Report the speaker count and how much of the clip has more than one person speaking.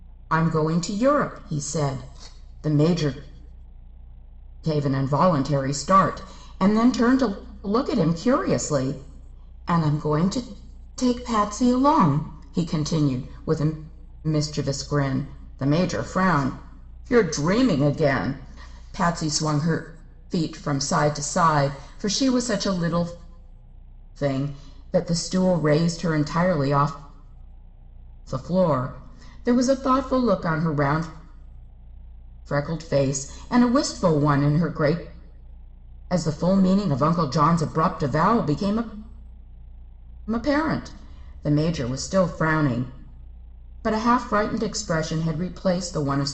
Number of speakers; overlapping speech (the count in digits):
1, no overlap